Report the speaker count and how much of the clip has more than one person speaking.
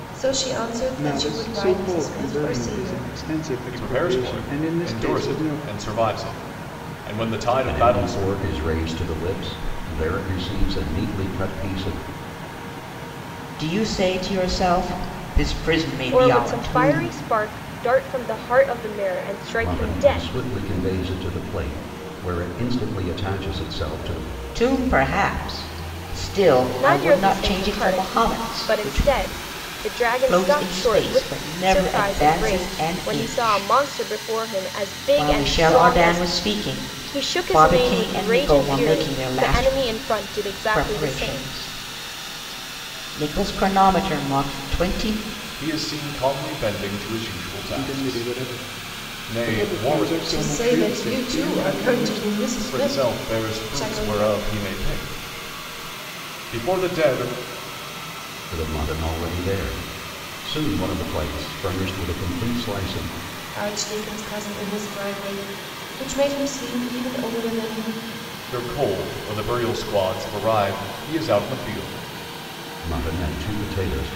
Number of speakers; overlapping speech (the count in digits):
6, about 31%